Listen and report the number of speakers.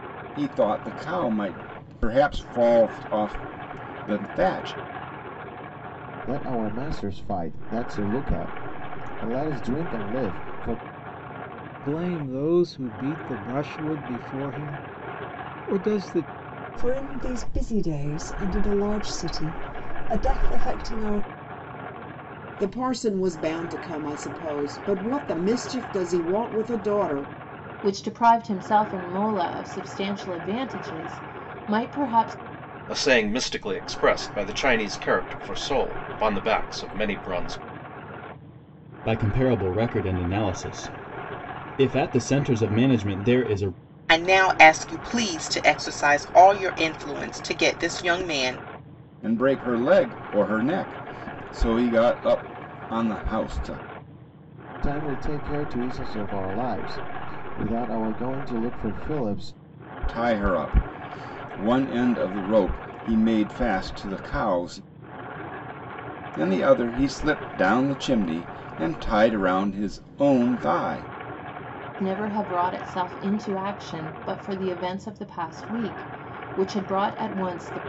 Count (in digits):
9